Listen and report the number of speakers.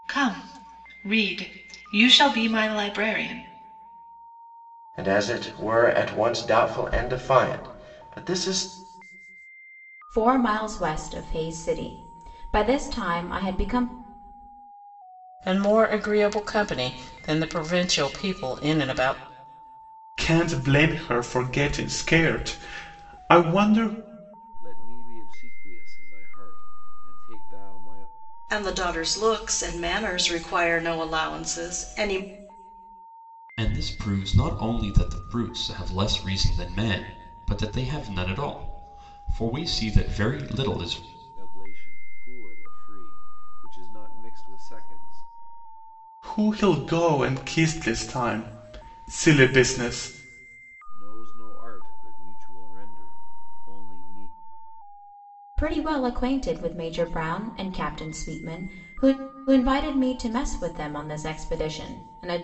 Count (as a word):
eight